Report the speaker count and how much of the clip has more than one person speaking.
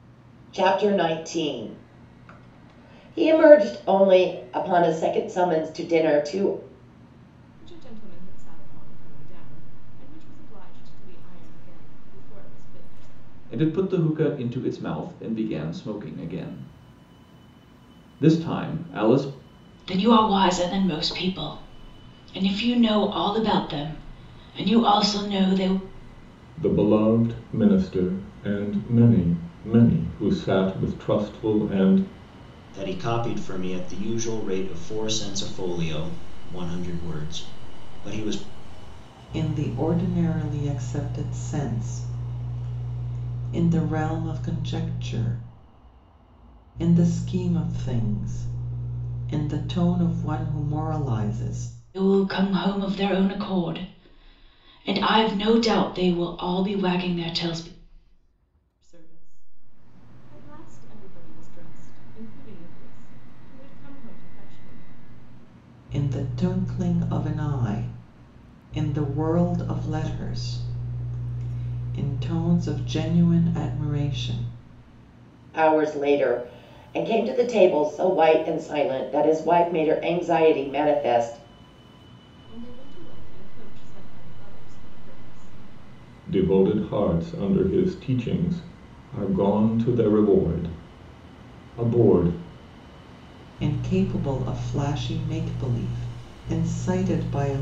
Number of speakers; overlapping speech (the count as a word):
seven, no overlap